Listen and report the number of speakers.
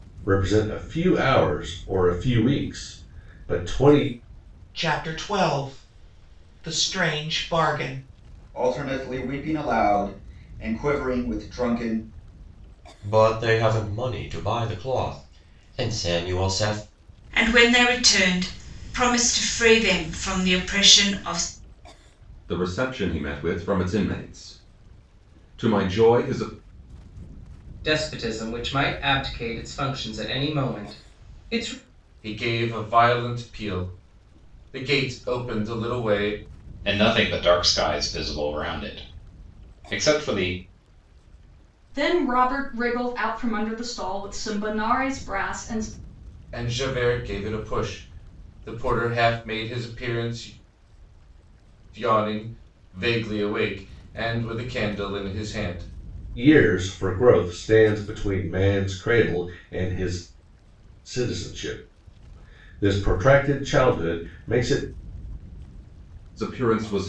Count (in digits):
10